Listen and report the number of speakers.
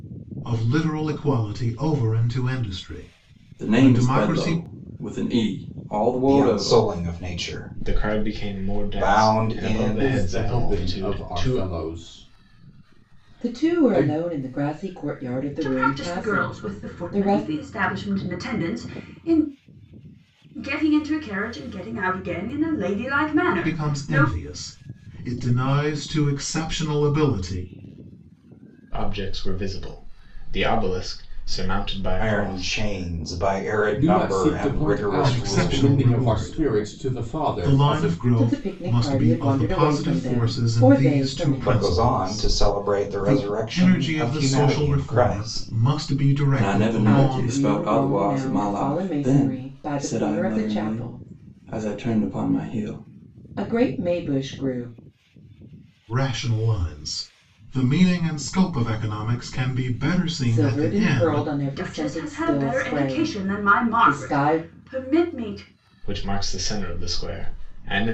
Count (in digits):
7